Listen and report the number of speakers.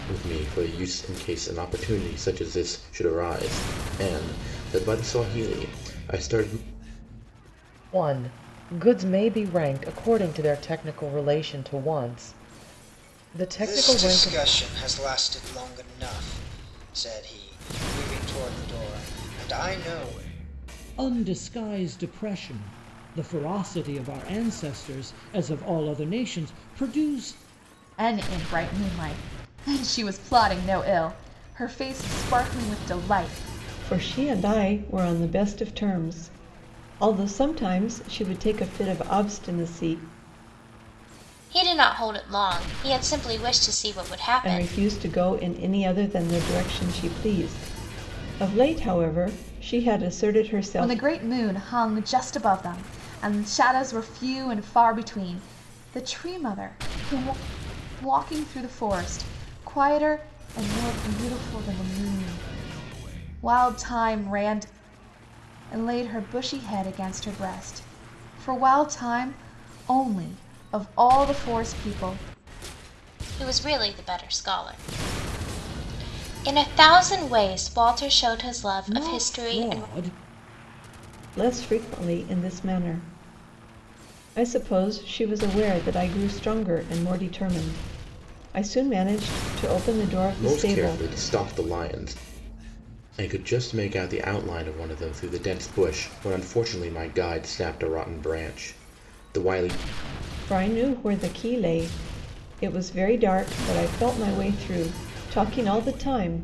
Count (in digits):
7